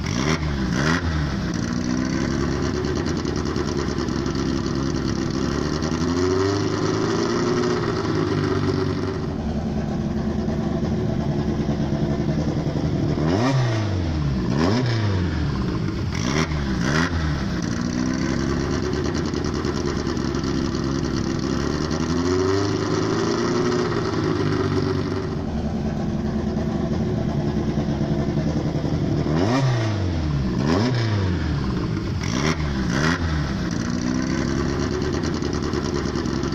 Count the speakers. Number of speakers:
zero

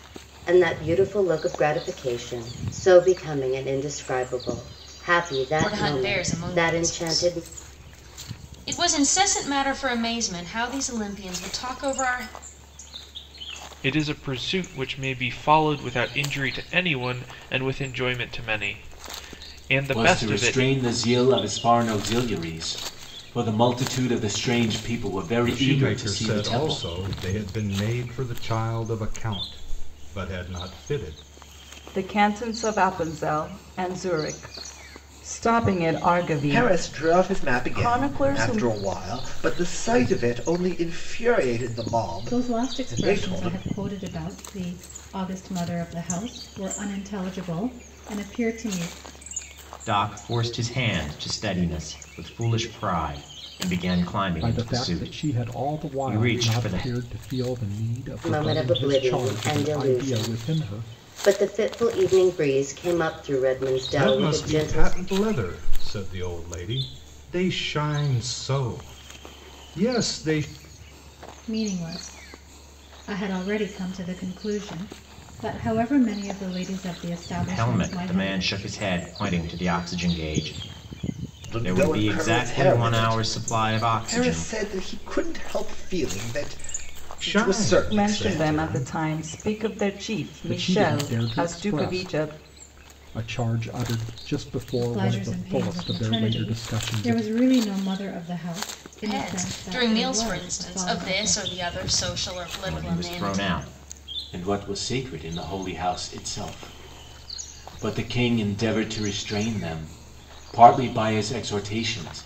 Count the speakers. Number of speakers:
ten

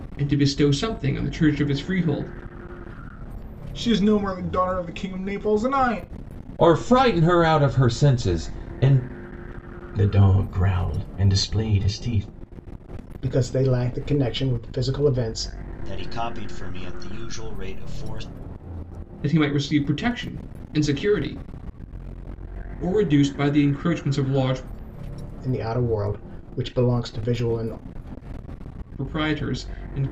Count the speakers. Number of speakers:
six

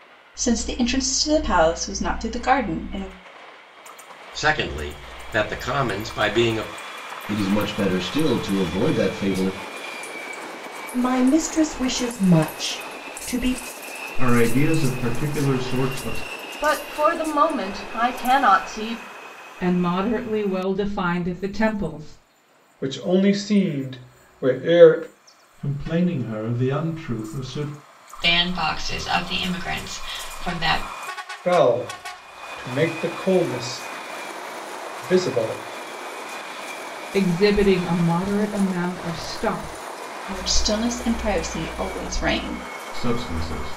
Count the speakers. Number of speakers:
ten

